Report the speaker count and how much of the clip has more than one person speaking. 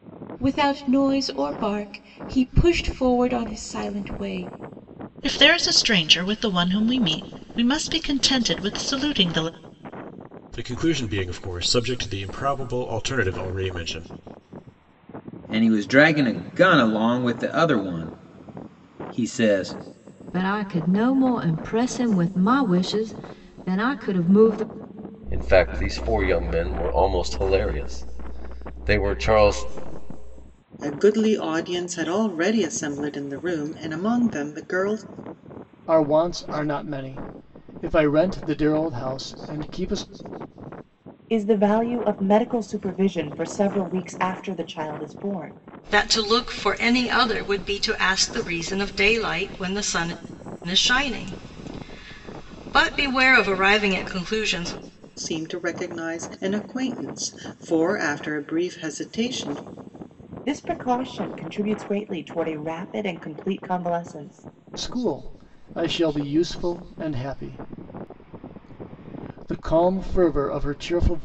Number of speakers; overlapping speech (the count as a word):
ten, no overlap